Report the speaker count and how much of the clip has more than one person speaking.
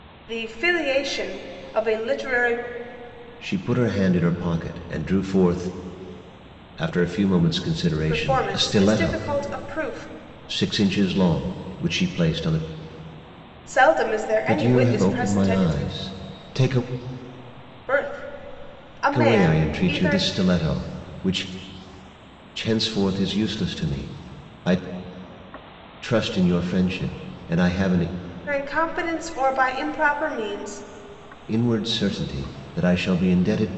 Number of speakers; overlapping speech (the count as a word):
two, about 11%